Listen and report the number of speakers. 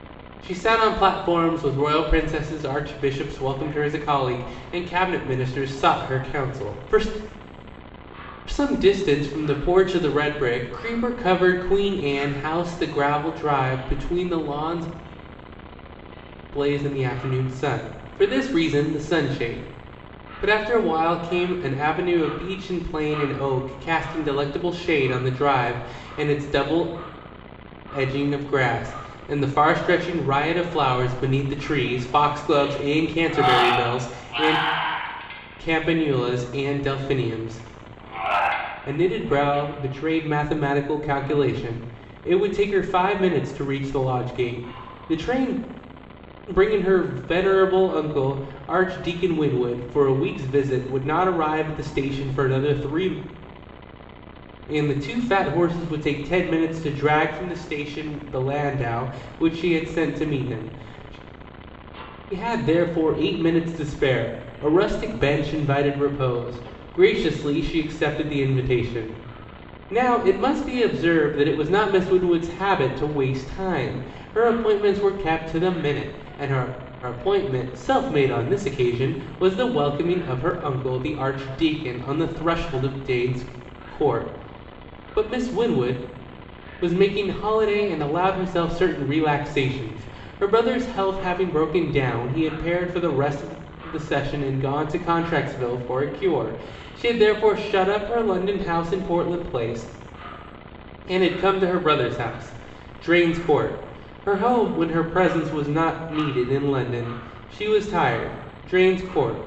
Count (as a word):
one